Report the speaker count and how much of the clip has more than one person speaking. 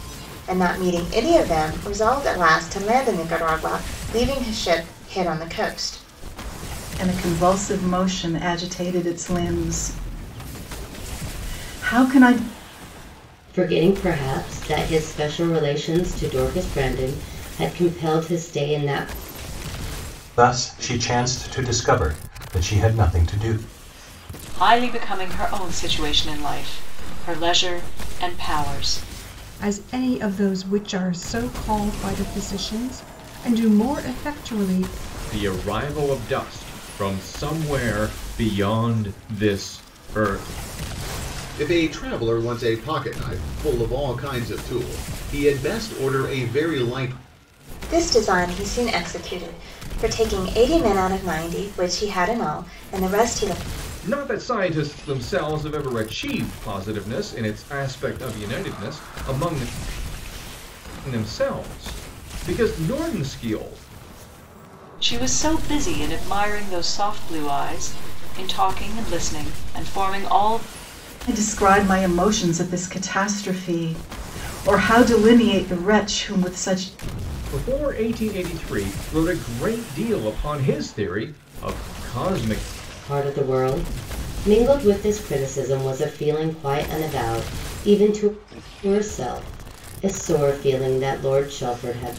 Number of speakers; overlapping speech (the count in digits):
8, no overlap